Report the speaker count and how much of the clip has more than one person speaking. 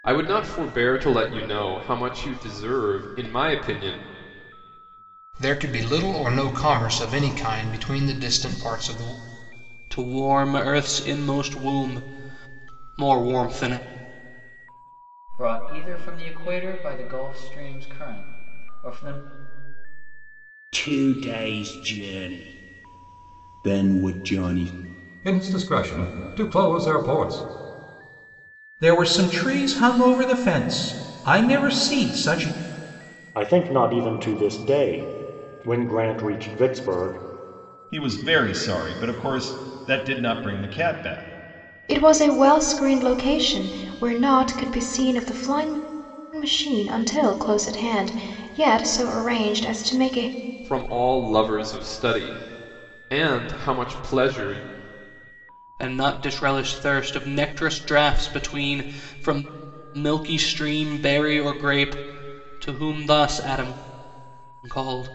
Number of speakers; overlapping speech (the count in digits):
10, no overlap